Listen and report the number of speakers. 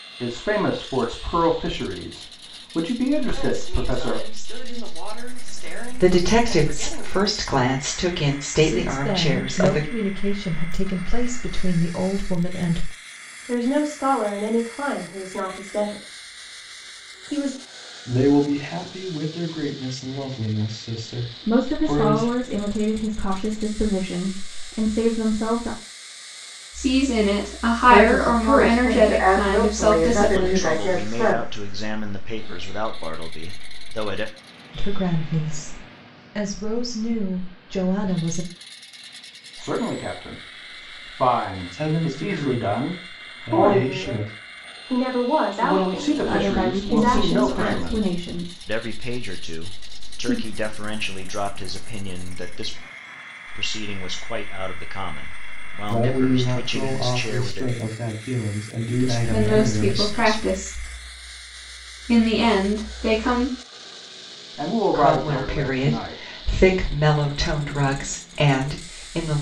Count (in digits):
10